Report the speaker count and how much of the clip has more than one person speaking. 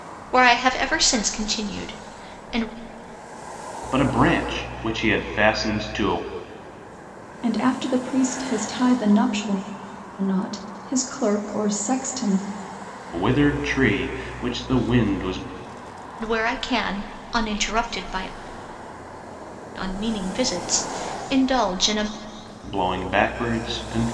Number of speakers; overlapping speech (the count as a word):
three, no overlap